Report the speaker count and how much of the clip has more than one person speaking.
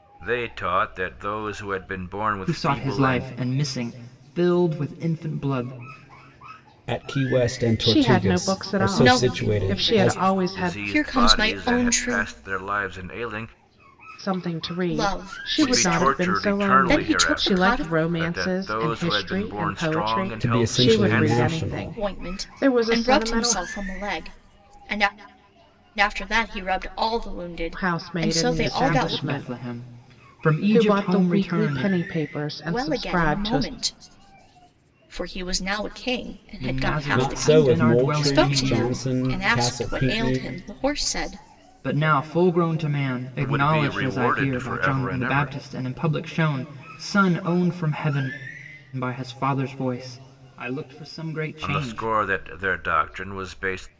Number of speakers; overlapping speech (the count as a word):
five, about 46%